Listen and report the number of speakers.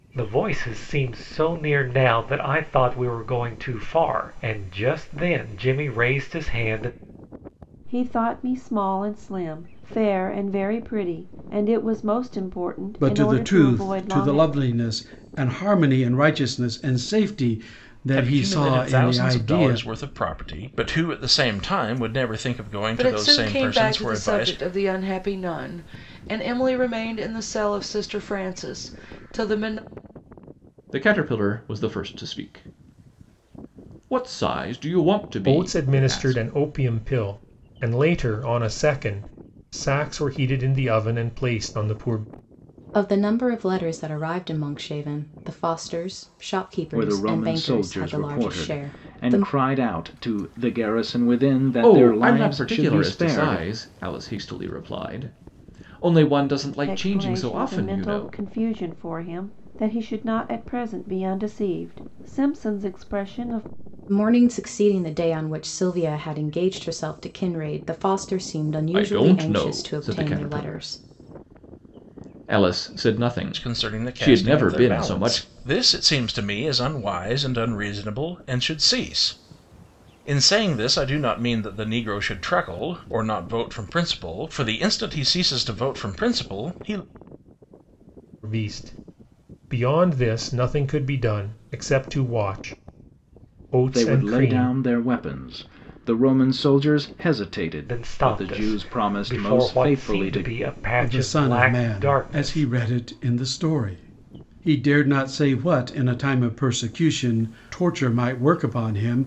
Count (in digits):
9